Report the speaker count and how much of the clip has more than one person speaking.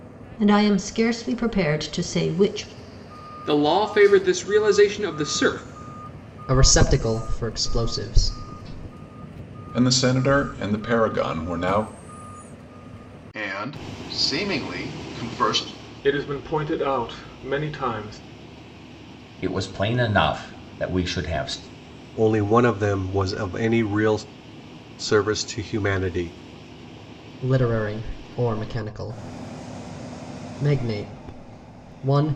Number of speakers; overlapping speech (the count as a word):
eight, no overlap